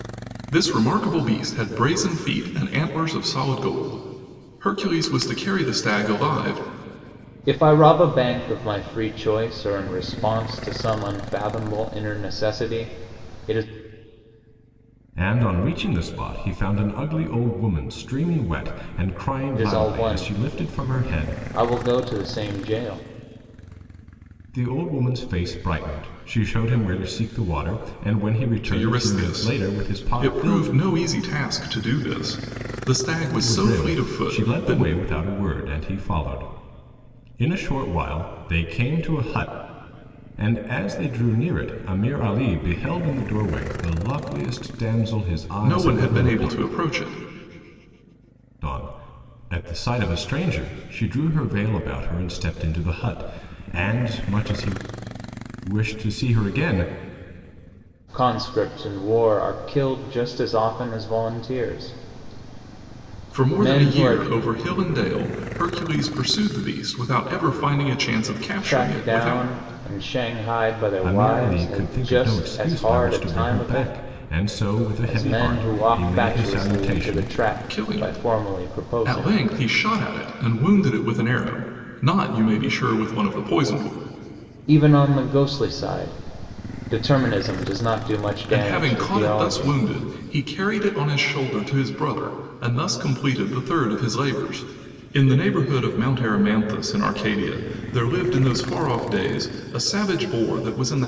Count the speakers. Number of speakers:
3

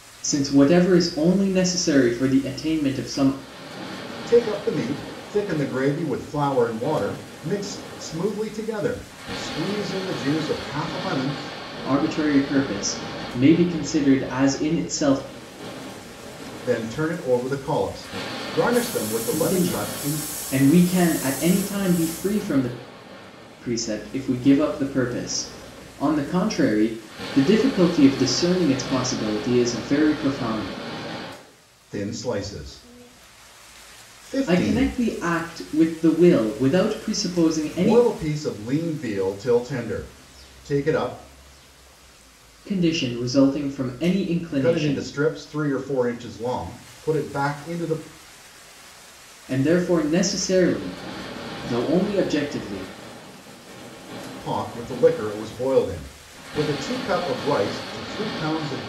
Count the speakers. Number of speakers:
2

